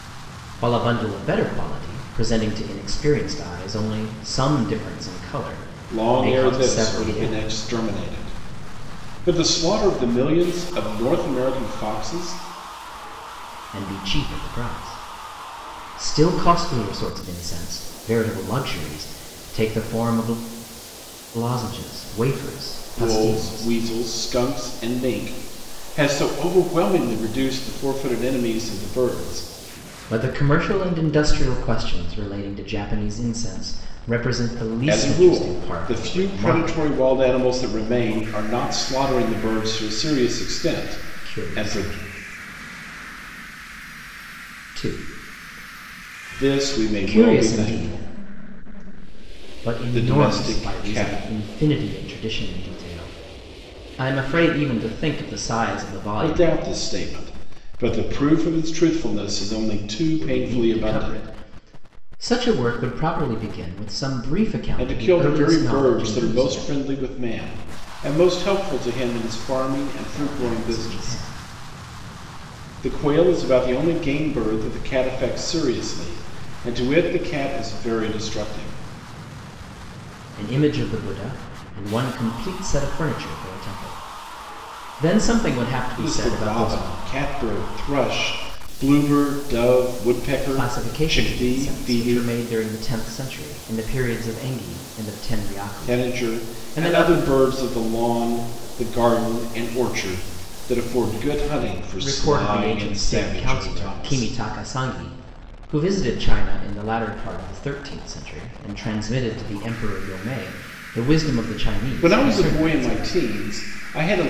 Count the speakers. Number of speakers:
2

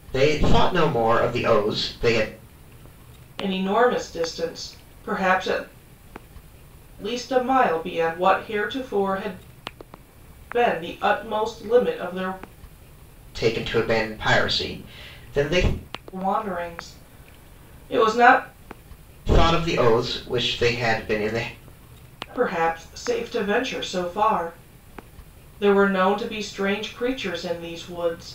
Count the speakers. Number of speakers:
2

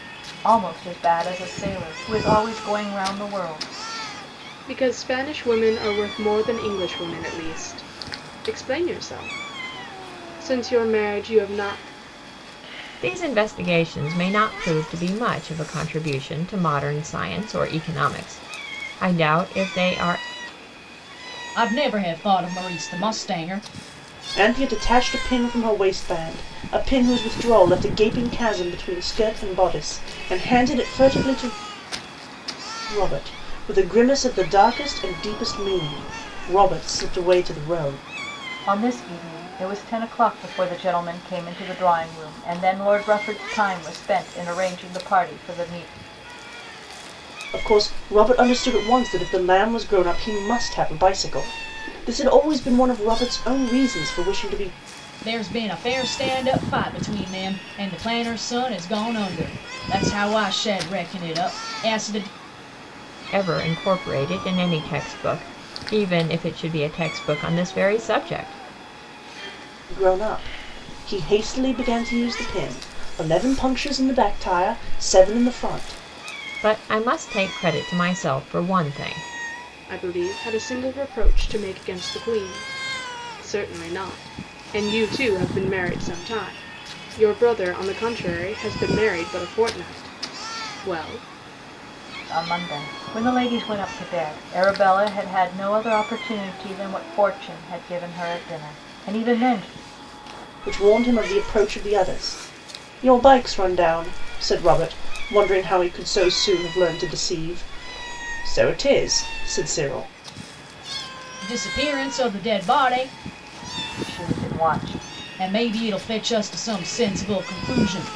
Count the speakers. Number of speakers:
5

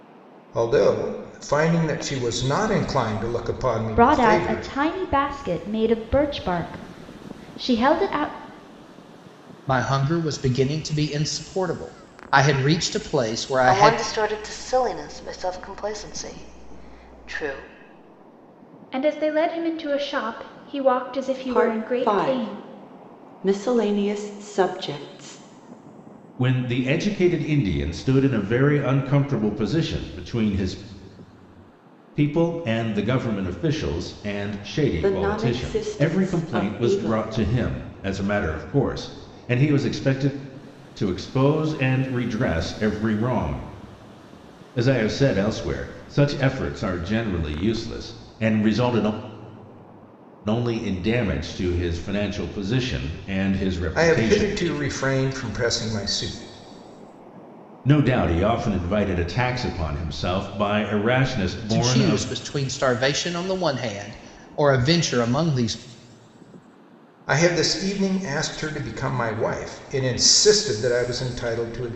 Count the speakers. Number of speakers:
7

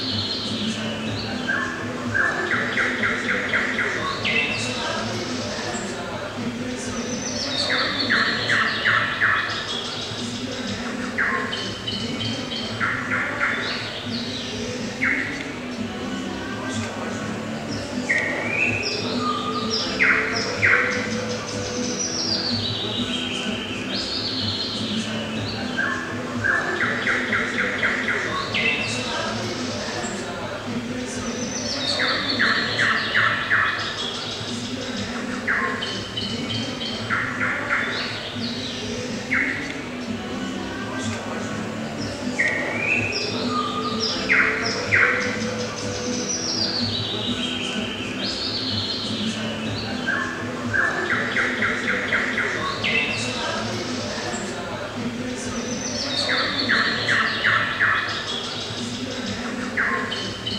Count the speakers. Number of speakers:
0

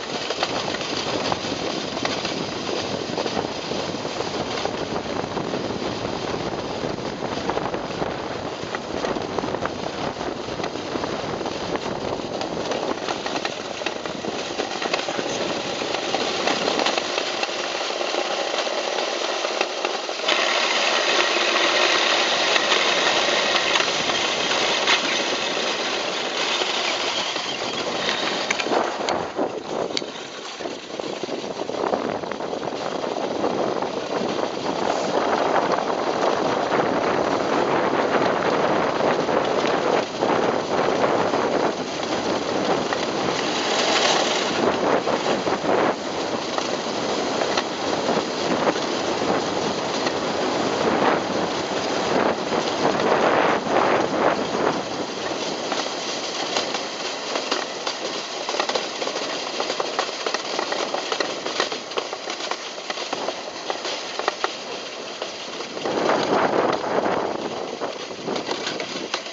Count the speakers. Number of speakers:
0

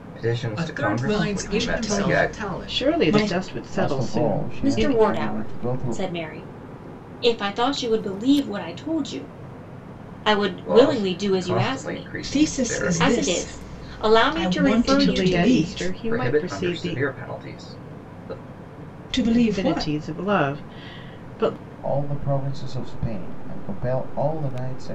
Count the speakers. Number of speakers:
6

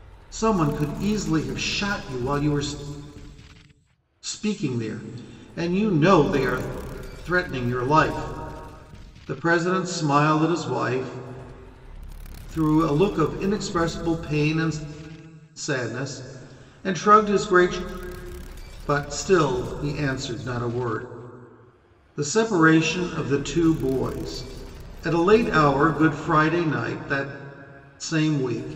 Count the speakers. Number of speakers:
1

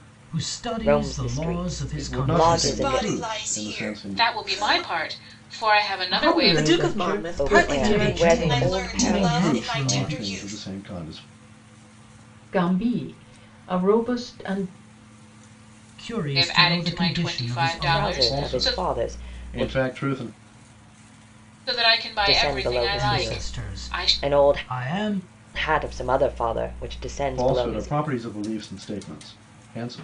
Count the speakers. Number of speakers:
7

